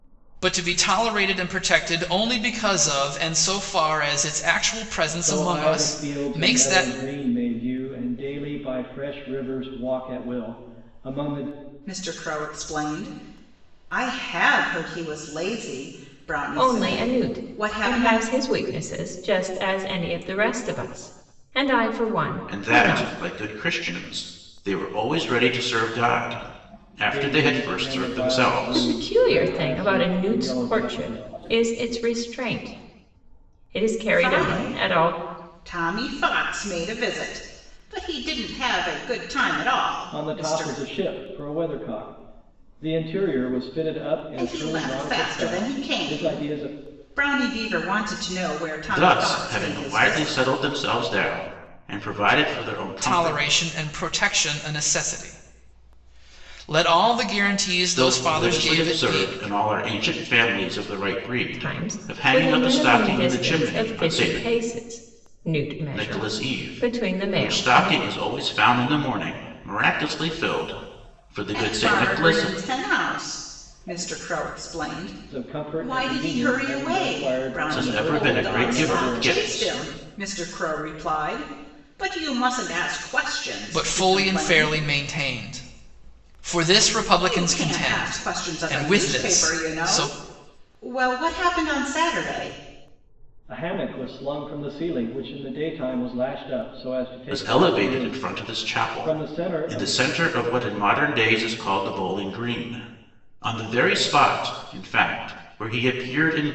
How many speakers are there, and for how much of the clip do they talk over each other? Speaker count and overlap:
five, about 32%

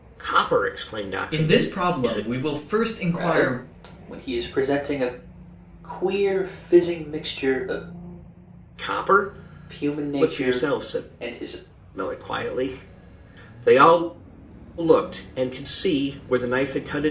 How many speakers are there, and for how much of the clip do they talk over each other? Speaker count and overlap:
three, about 18%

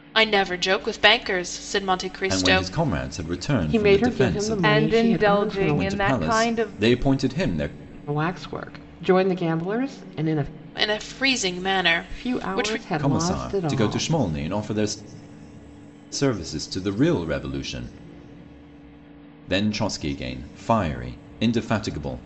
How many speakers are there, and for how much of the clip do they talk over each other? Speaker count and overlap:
four, about 24%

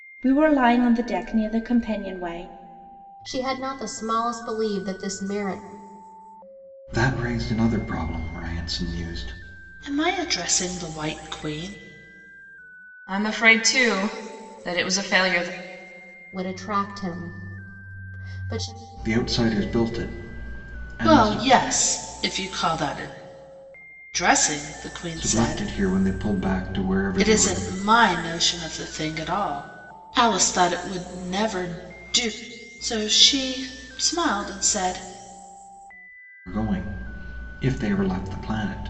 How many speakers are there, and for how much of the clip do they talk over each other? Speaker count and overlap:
five, about 4%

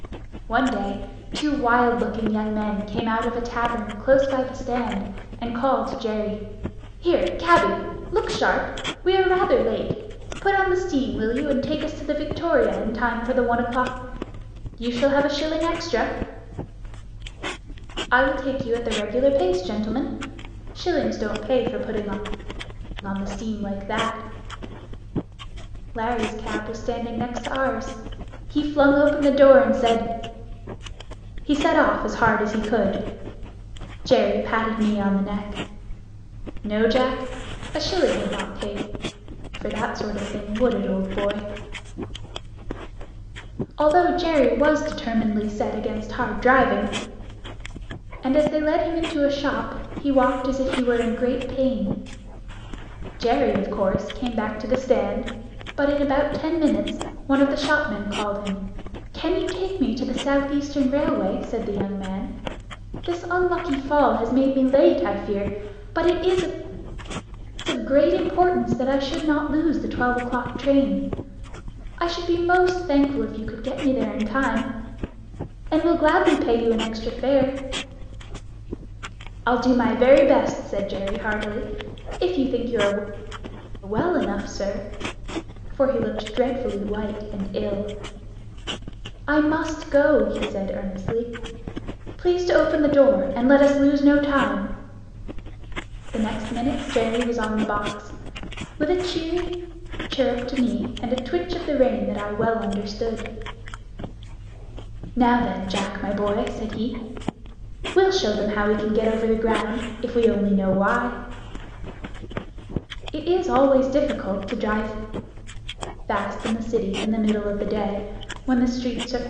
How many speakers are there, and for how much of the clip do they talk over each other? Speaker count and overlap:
one, no overlap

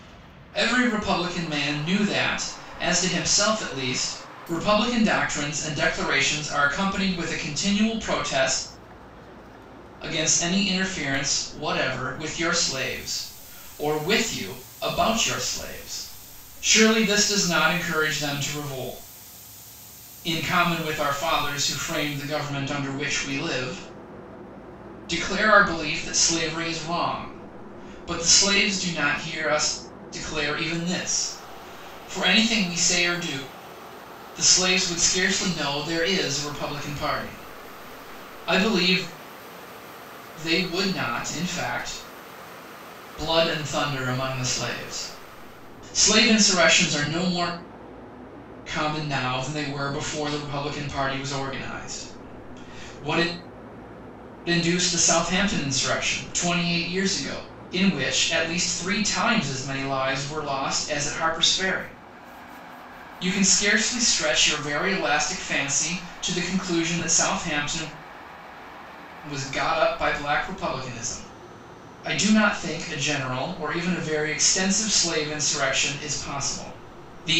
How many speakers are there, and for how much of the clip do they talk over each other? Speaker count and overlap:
one, no overlap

